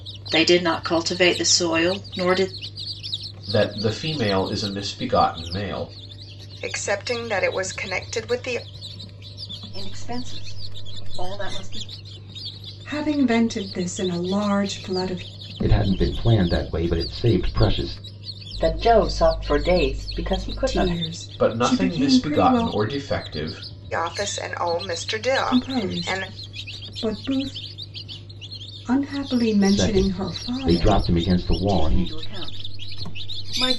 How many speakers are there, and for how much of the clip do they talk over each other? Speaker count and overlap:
7, about 13%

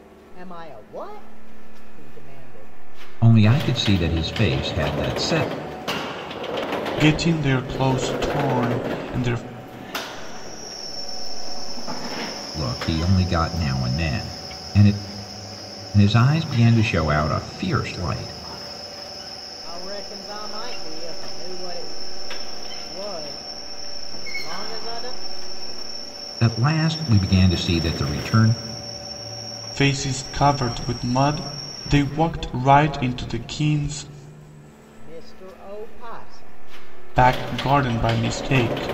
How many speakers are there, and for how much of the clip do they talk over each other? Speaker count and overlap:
3, no overlap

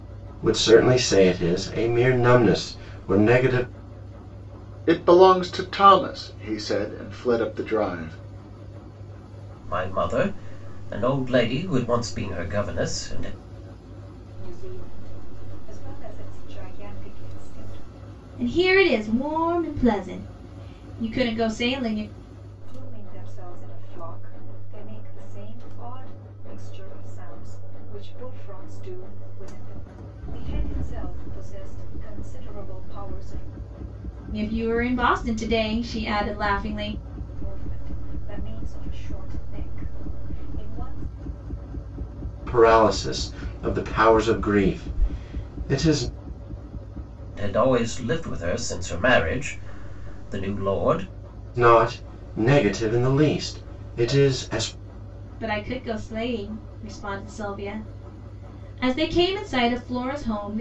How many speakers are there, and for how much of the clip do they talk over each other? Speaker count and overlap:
5, no overlap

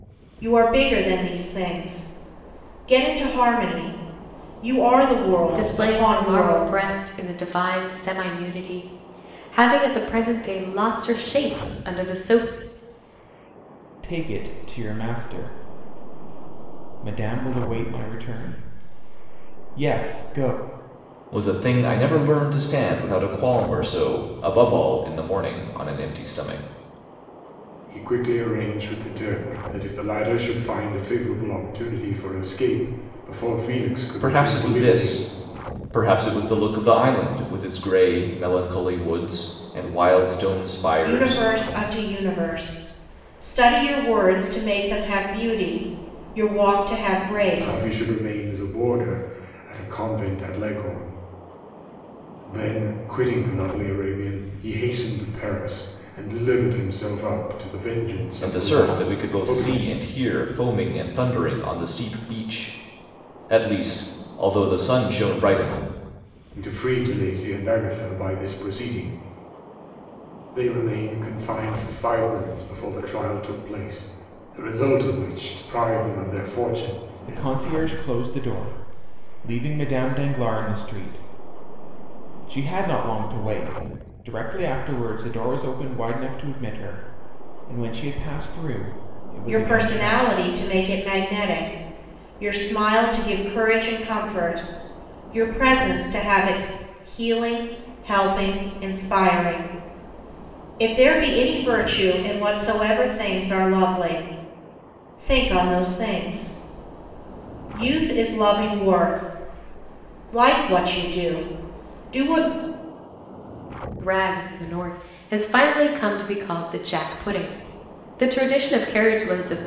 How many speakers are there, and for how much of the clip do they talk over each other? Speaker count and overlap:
5, about 5%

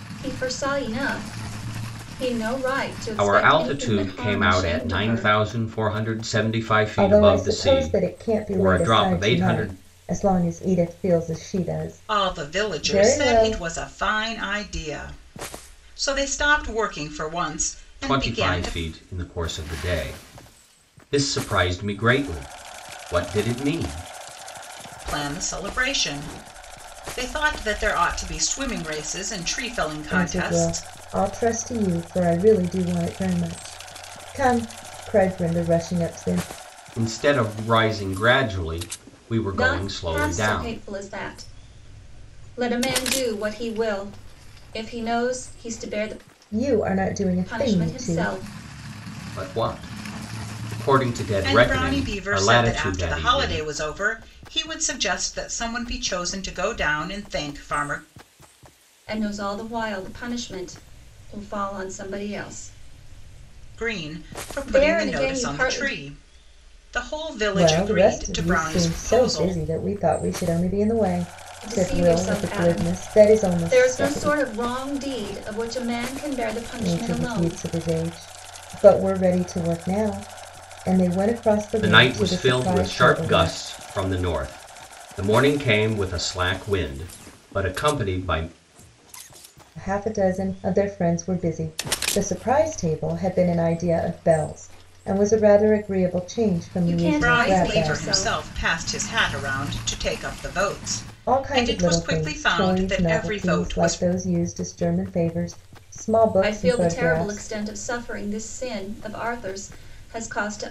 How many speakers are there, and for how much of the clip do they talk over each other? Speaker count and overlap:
4, about 25%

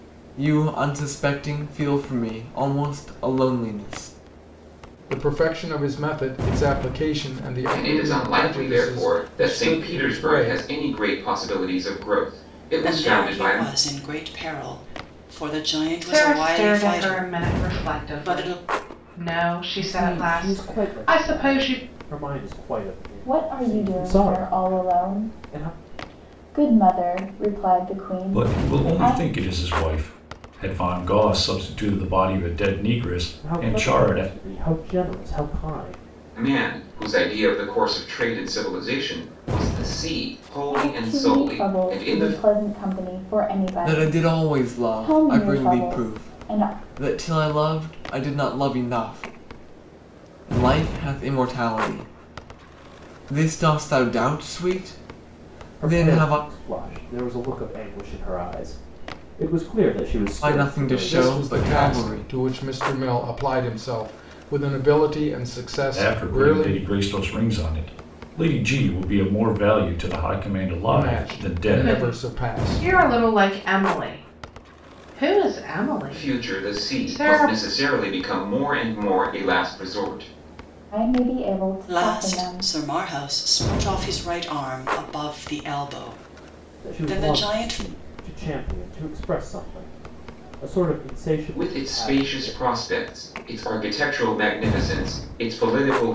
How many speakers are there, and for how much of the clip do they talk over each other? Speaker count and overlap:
8, about 28%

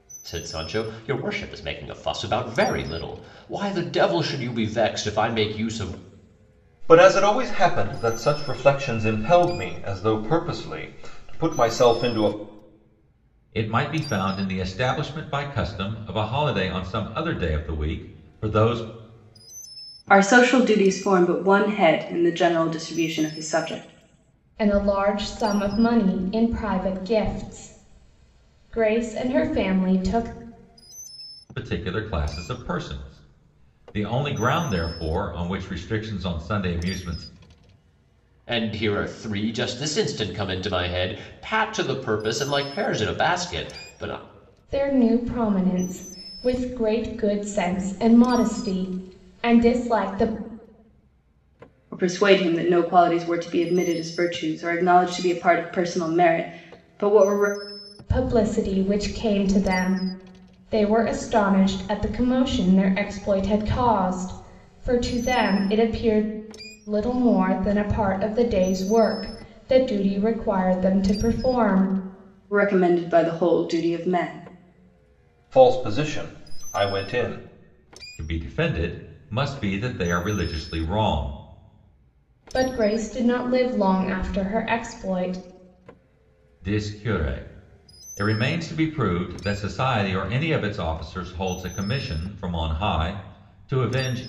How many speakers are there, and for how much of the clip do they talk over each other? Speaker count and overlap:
5, no overlap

